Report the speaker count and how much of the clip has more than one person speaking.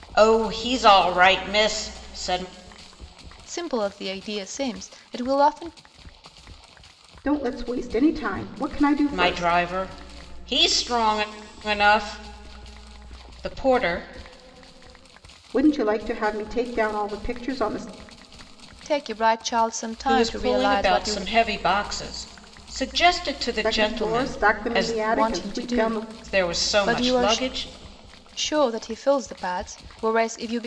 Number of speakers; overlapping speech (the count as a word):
three, about 17%